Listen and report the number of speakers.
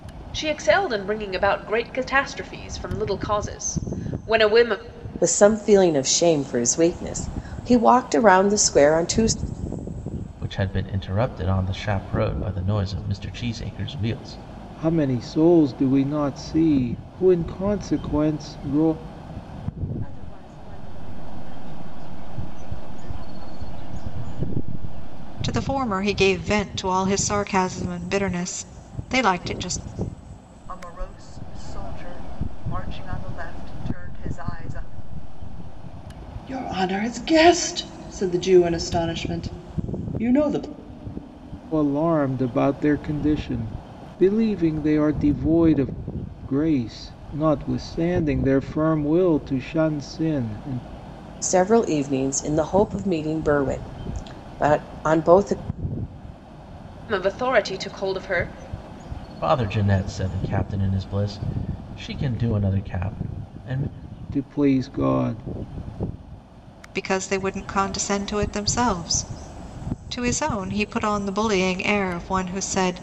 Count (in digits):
8